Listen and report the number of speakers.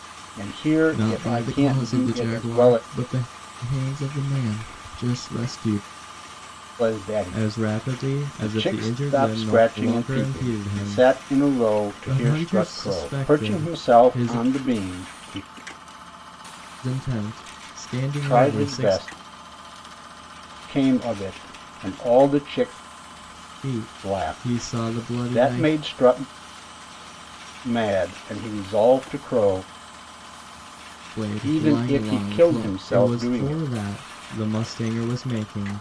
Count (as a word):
two